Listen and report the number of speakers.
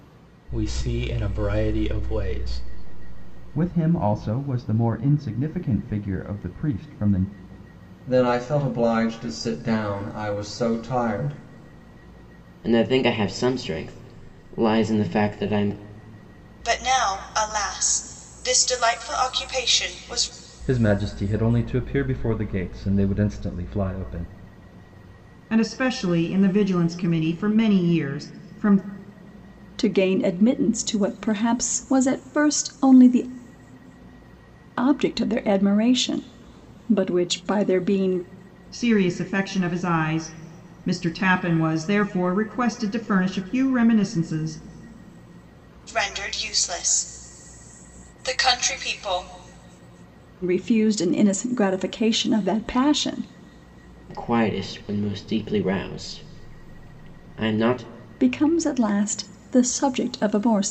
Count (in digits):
8